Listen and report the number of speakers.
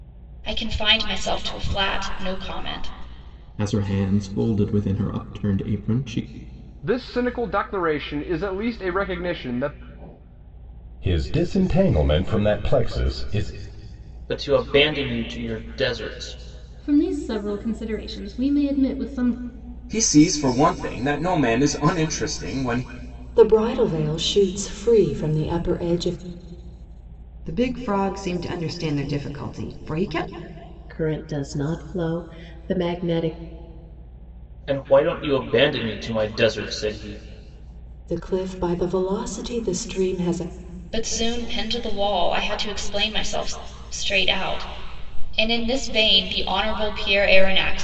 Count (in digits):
10